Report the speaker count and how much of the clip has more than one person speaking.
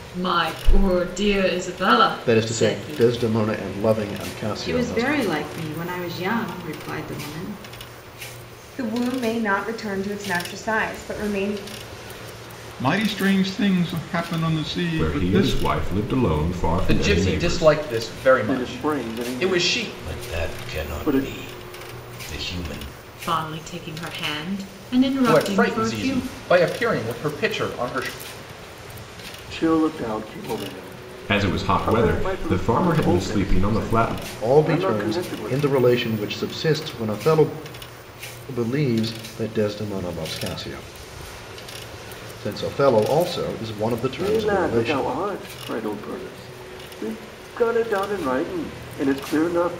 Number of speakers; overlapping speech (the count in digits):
9, about 24%